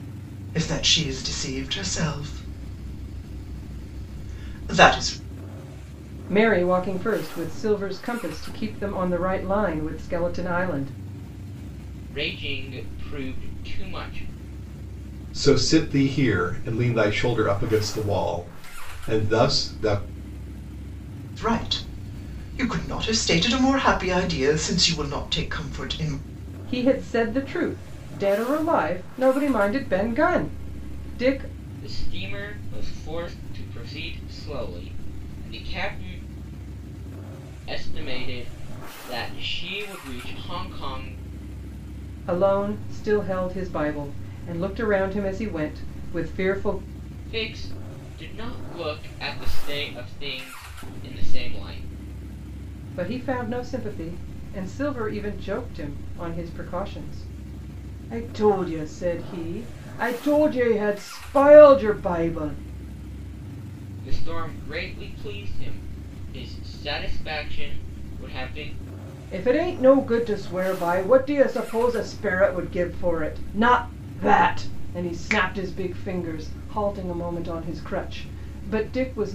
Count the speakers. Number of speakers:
4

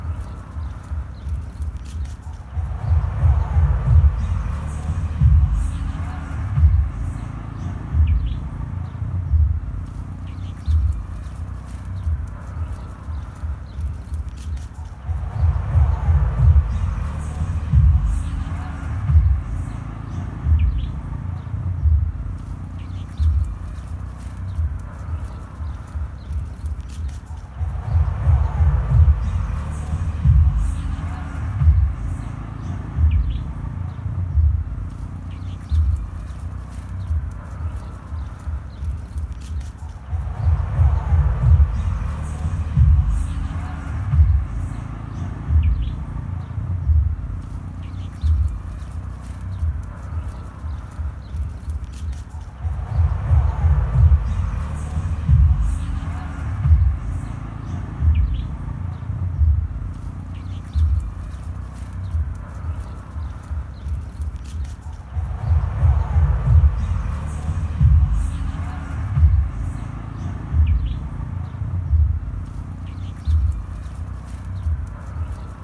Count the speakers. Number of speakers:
0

